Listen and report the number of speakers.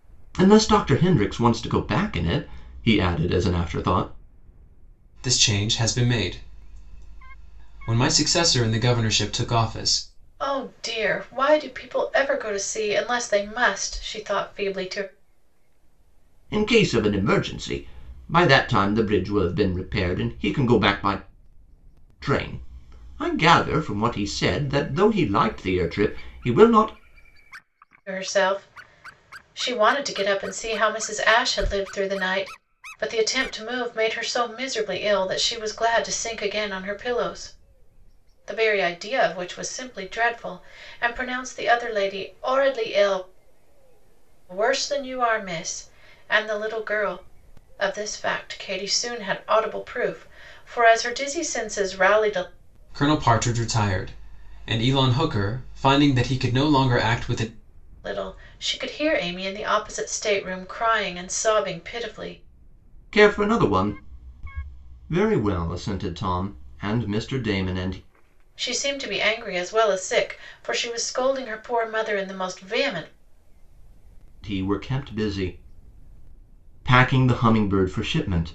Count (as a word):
three